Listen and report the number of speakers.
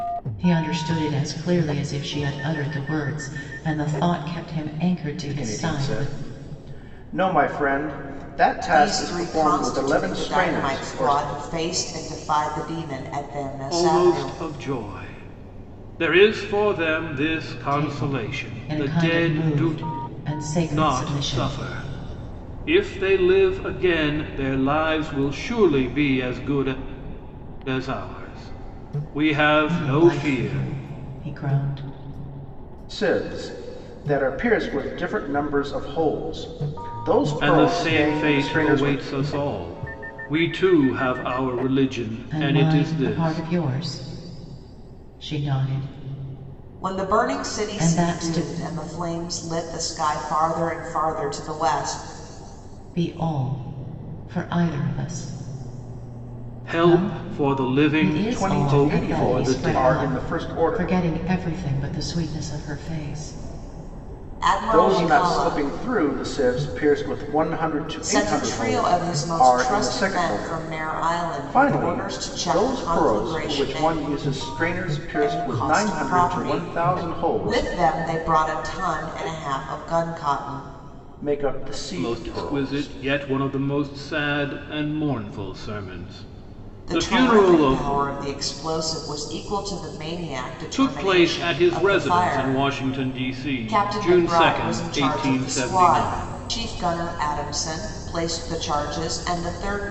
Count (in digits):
4